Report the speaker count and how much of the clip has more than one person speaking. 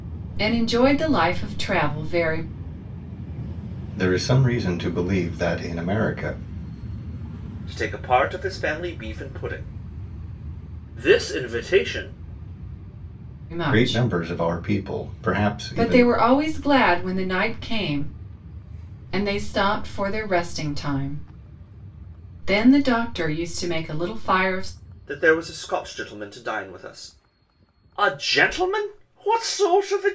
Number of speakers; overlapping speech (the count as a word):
three, about 3%